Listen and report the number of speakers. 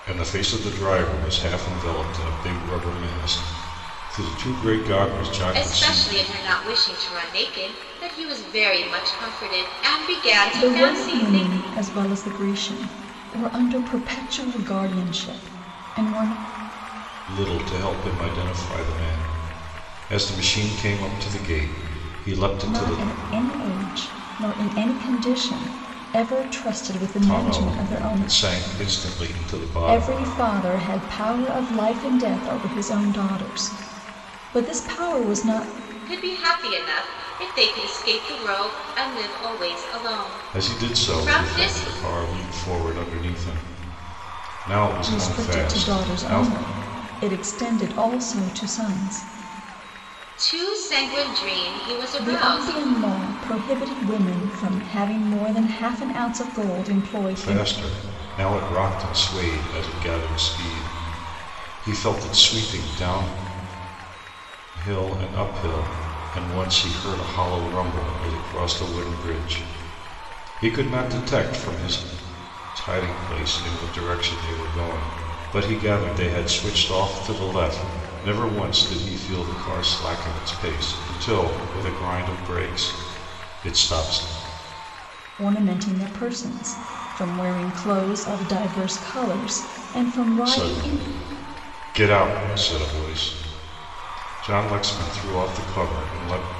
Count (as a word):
three